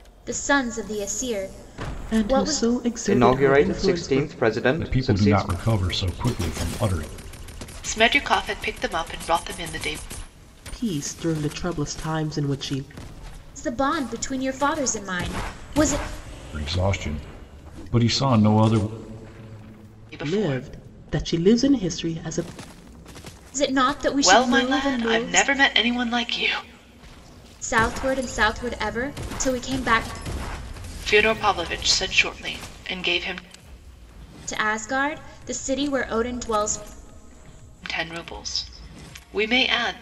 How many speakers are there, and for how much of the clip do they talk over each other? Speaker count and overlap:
5, about 11%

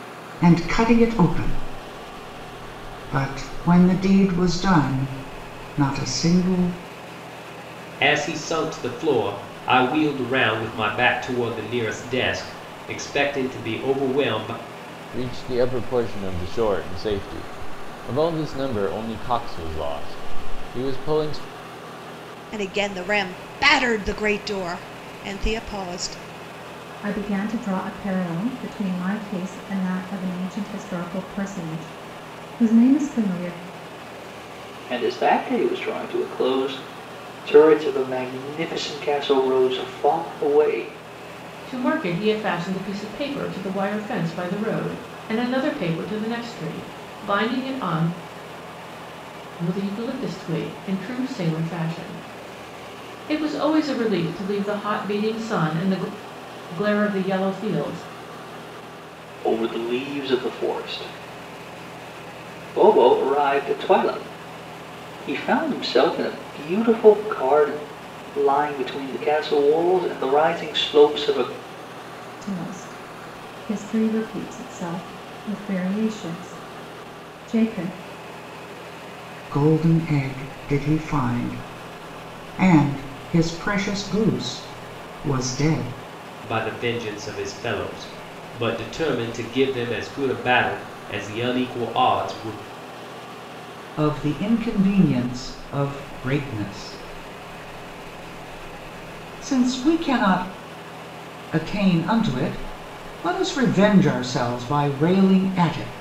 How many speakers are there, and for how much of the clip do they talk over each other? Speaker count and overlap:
7, no overlap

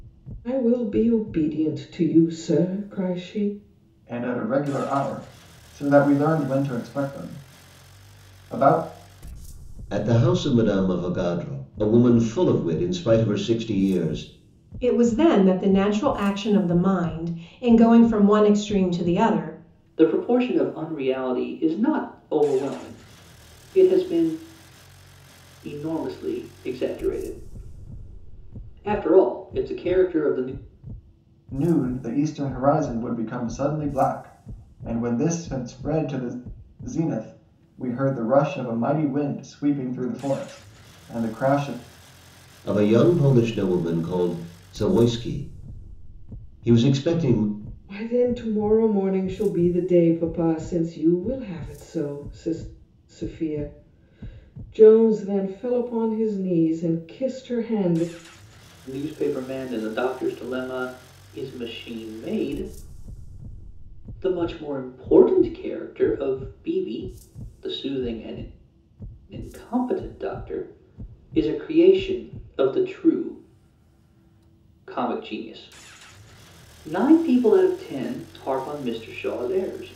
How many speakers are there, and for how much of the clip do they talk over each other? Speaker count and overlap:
5, no overlap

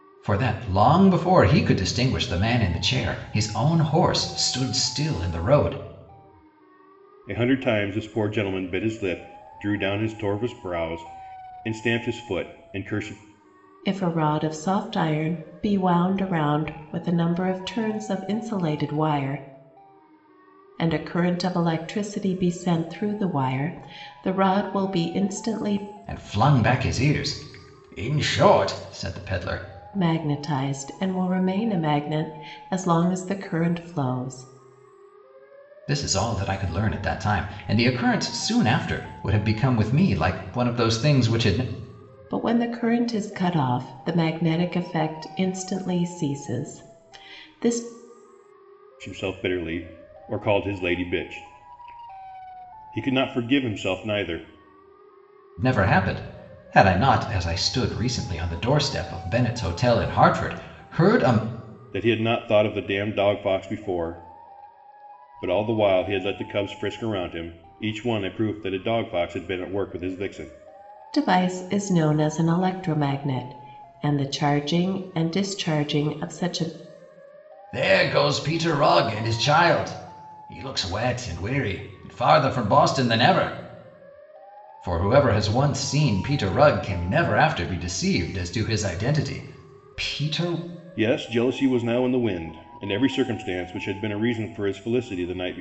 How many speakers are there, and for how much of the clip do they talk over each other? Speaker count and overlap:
3, no overlap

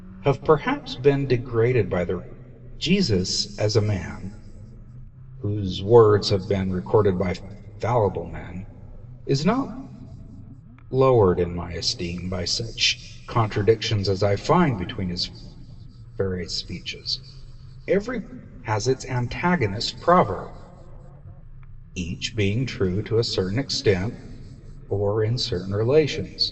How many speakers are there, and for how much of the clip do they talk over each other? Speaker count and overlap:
1, no overlap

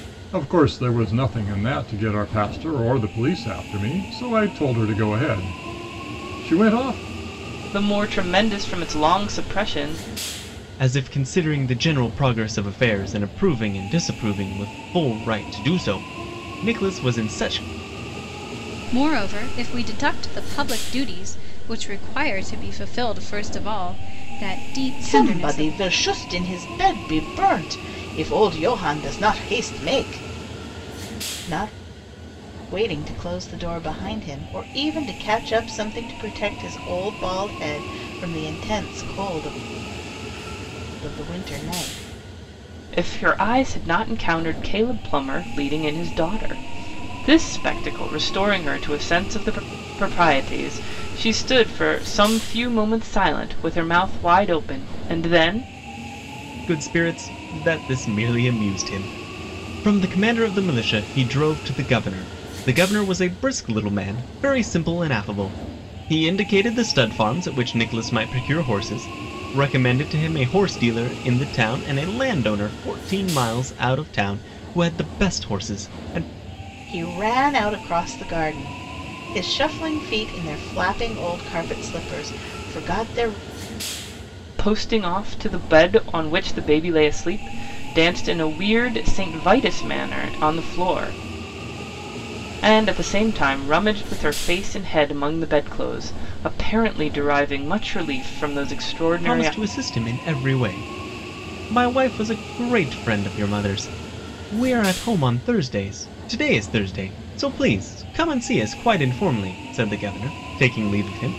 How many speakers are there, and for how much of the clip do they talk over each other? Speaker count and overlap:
5, about 1%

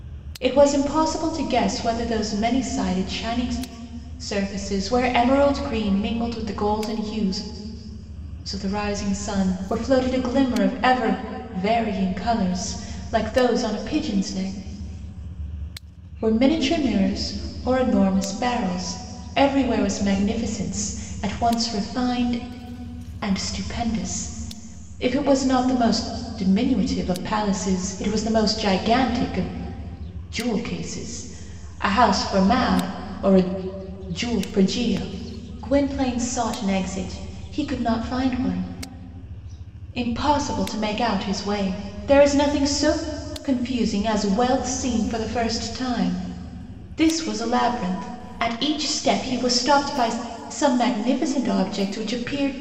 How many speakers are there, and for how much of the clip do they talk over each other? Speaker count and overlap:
1, no overlap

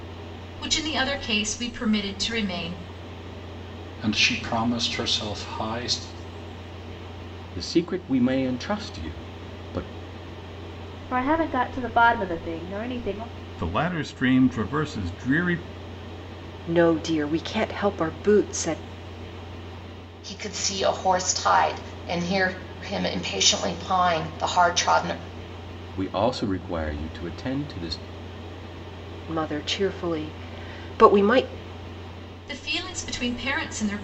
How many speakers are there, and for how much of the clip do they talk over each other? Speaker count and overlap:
7, no overlap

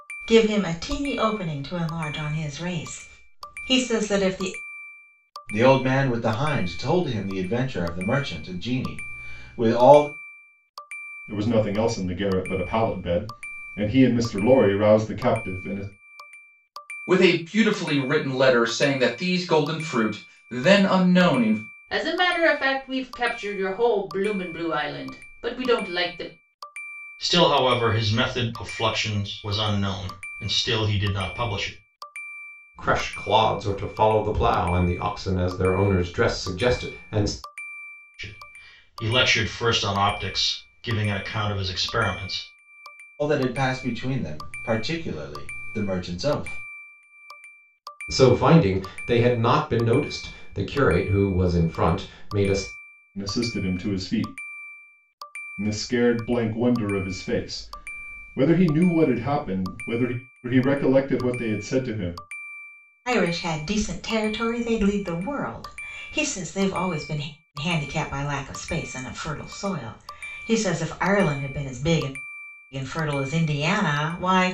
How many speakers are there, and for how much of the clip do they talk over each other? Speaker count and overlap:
7, no overlap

